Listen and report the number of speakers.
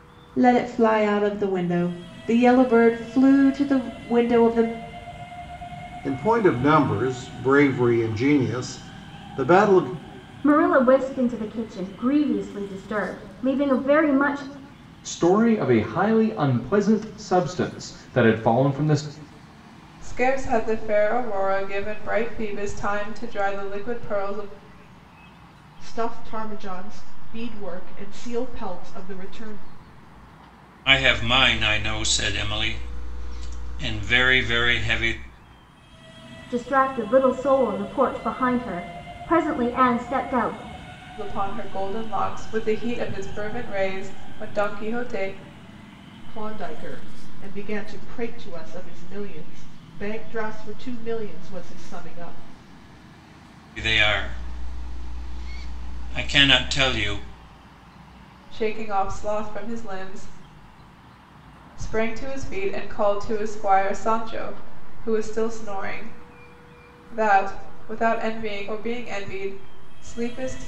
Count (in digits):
7